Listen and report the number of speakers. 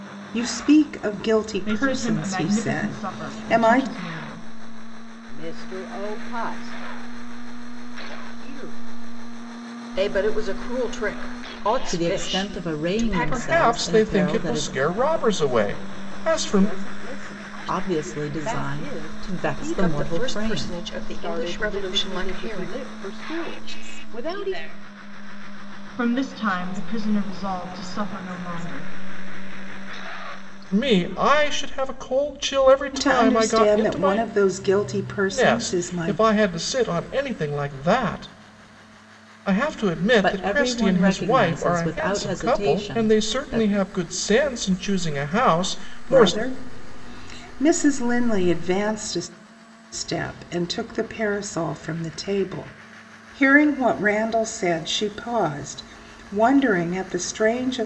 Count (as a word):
seven